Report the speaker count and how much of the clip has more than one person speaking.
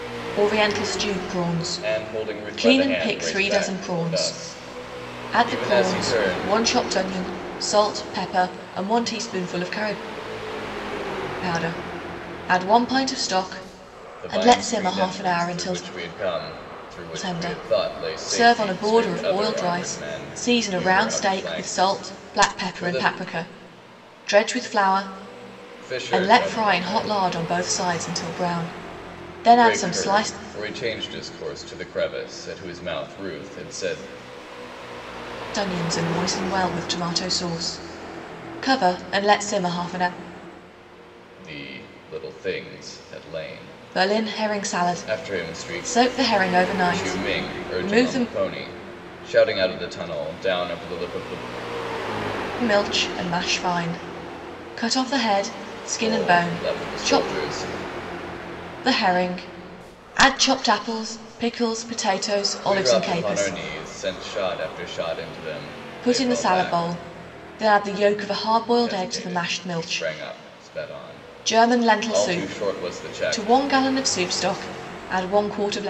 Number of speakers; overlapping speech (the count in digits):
2, about 31%